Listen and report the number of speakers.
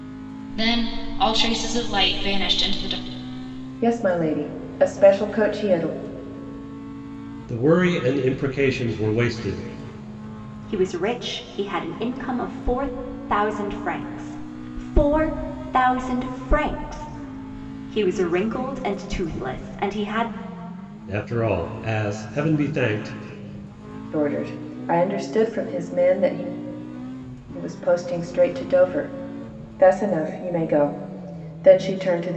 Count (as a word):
four